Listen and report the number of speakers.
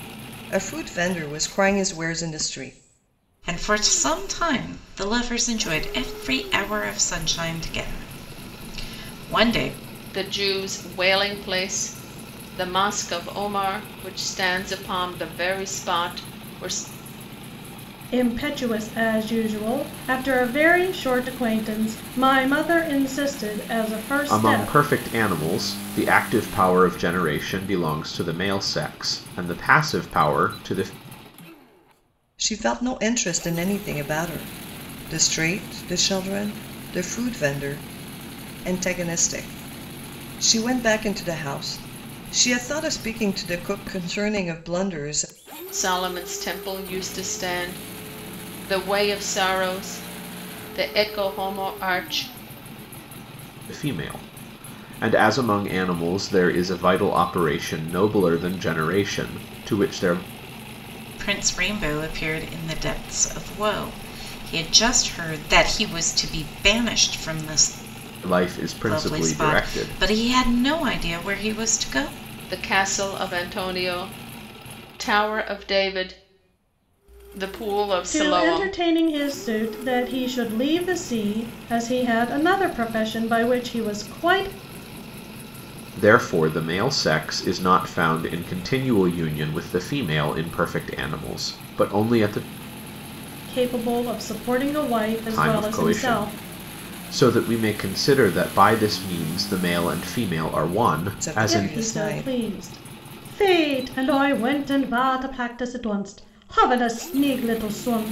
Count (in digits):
5